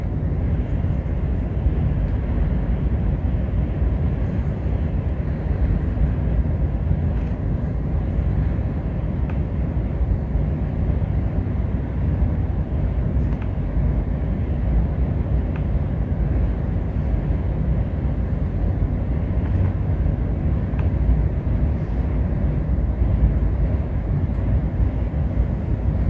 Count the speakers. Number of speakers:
0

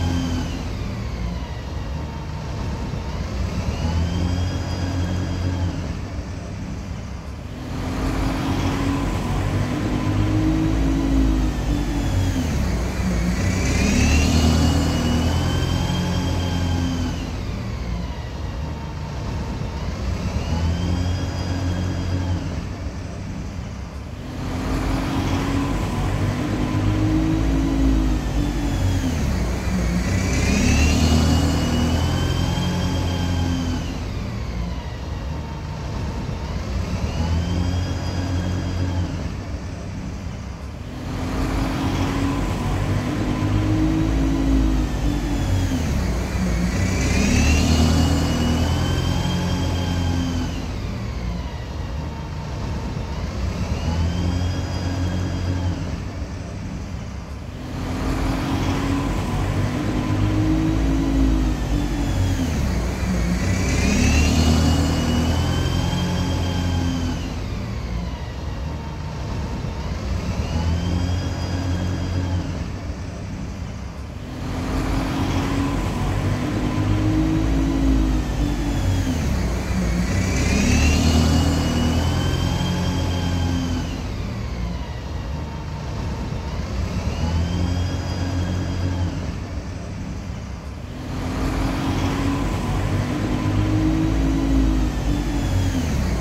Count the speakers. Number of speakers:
0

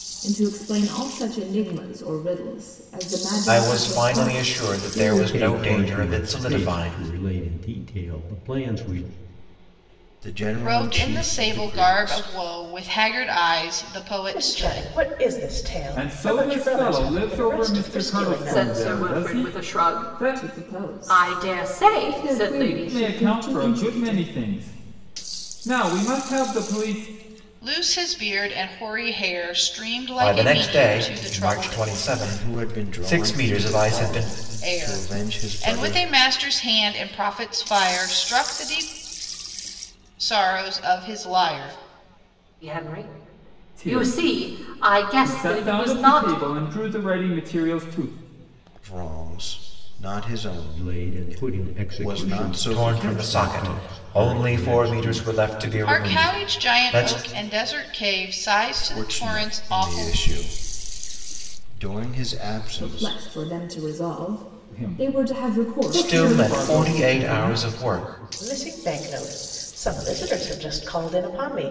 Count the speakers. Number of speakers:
8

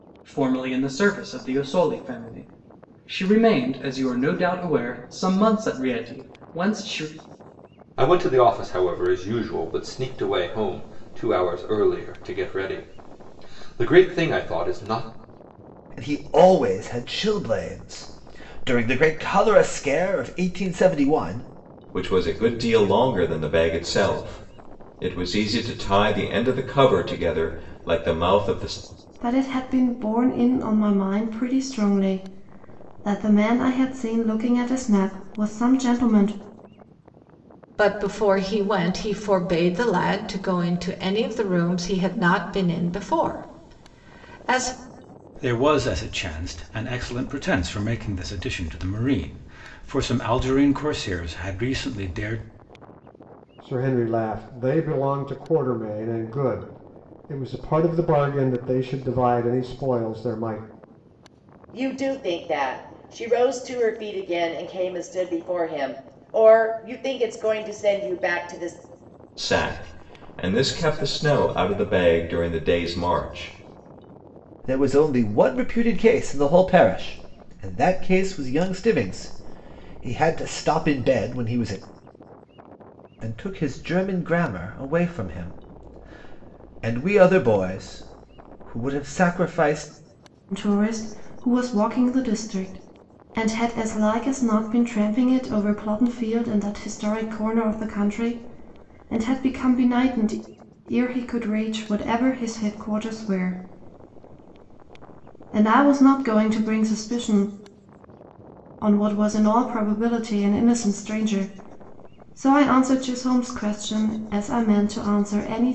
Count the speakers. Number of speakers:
9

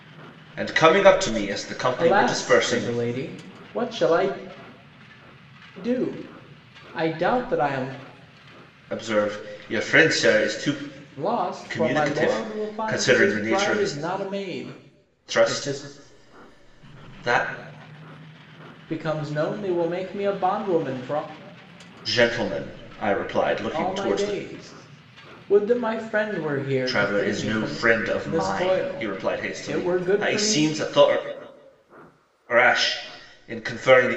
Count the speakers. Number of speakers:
2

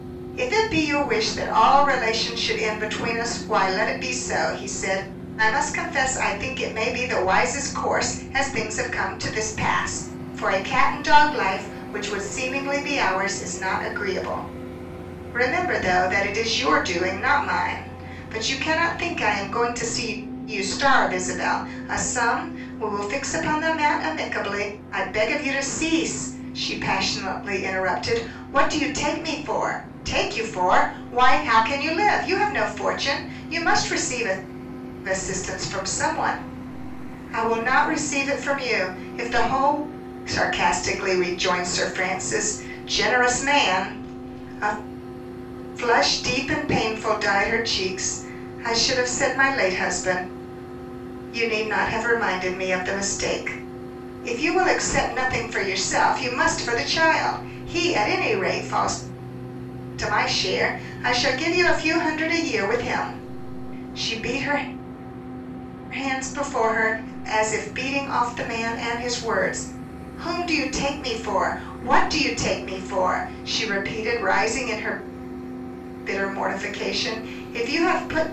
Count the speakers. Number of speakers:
1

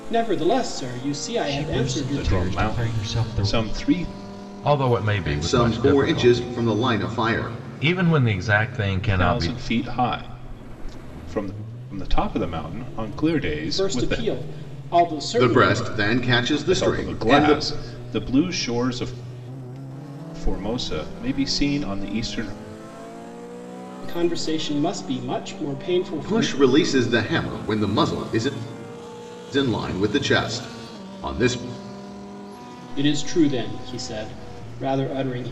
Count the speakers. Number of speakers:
5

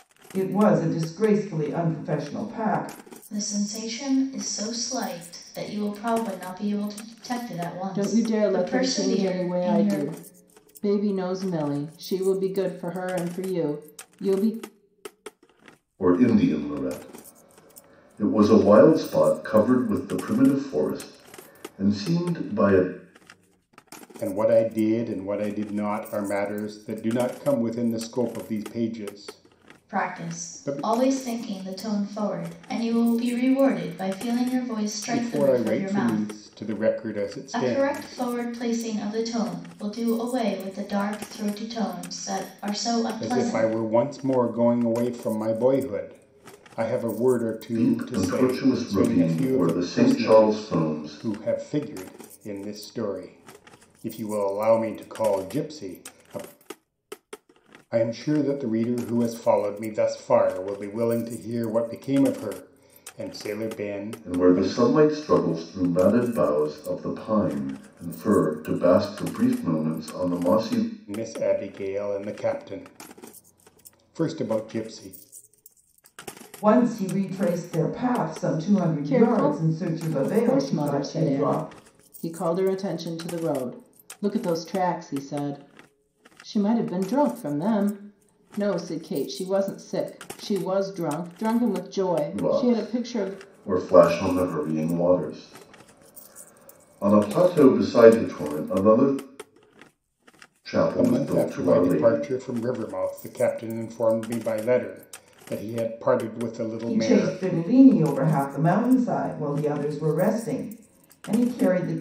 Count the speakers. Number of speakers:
5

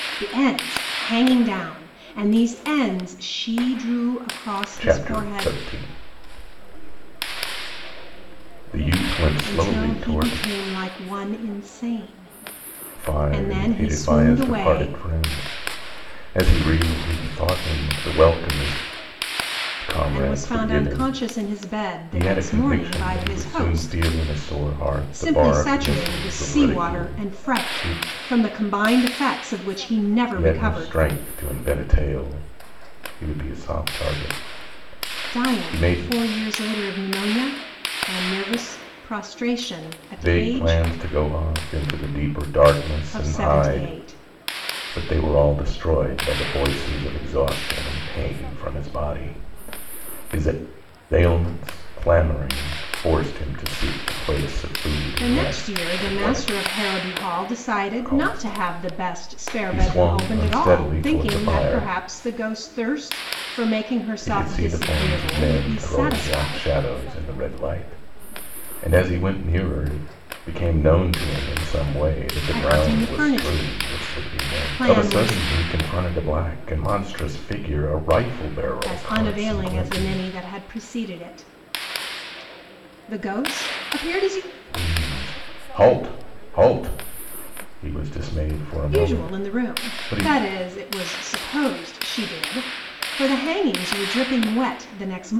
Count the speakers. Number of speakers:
2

